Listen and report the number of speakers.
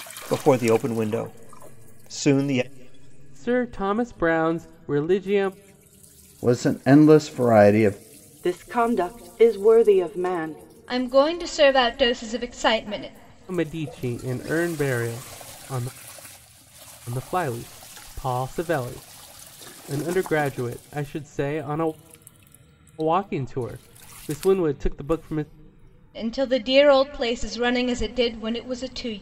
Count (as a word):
five